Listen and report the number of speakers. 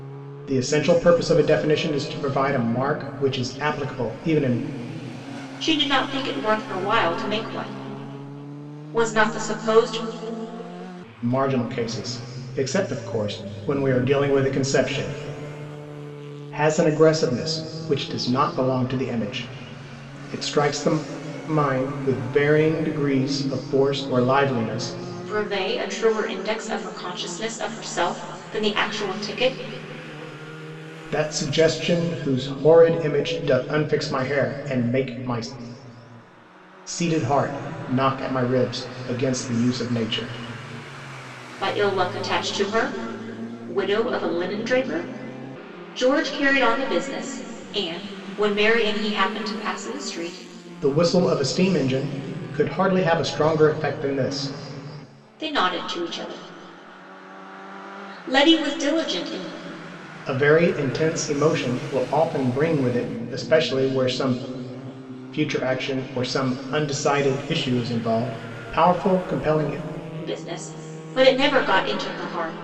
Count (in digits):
2